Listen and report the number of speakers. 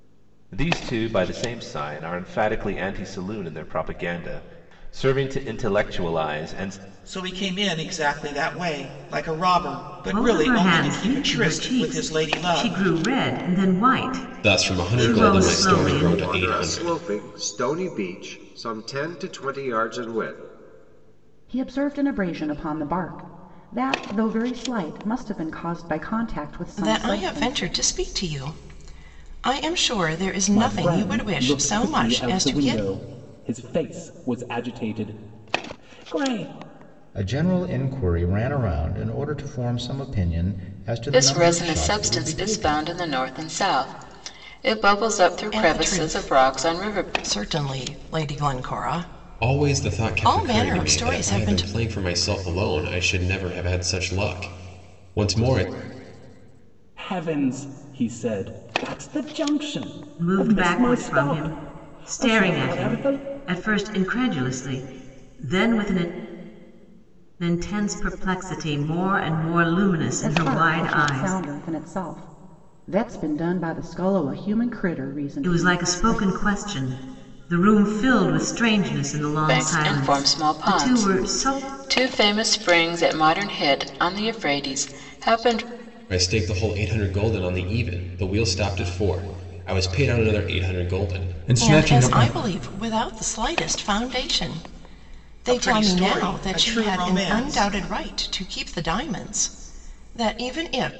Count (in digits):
10